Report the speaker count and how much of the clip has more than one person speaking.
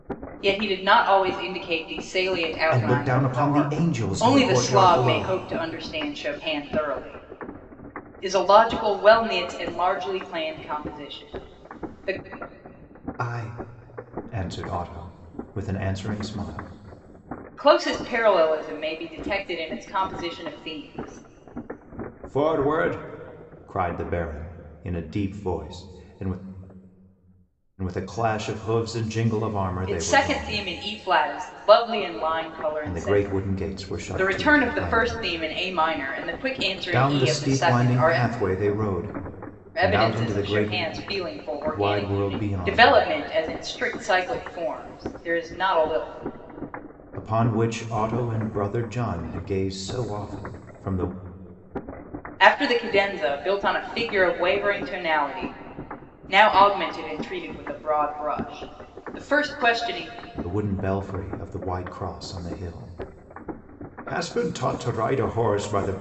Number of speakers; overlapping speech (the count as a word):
two, about 13%